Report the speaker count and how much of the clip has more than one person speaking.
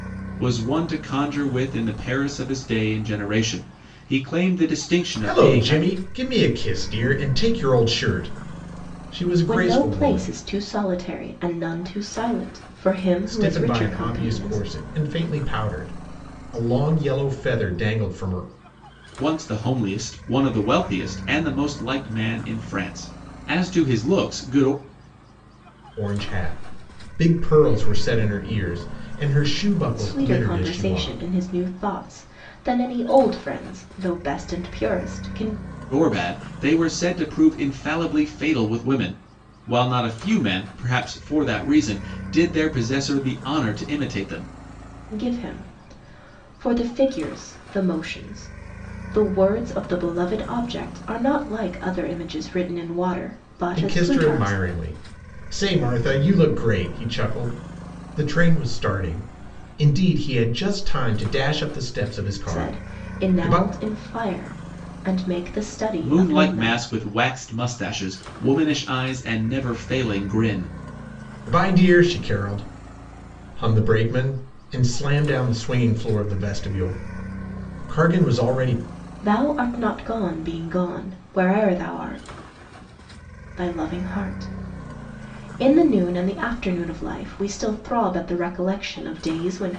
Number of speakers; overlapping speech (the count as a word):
three, about 8%